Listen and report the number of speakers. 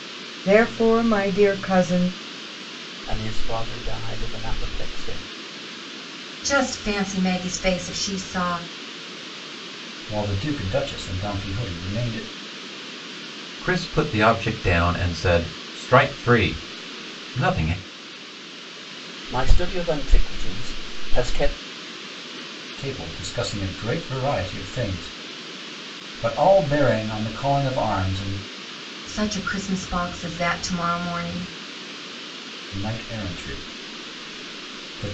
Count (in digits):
5